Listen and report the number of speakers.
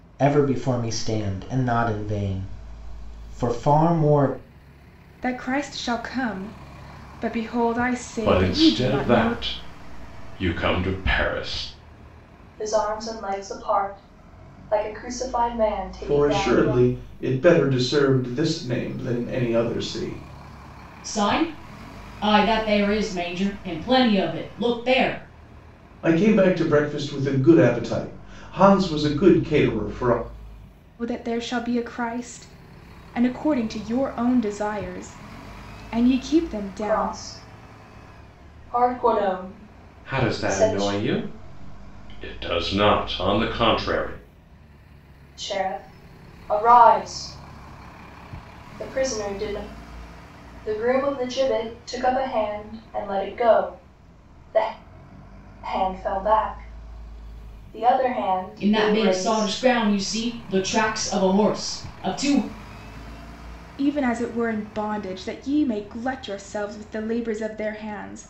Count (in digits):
6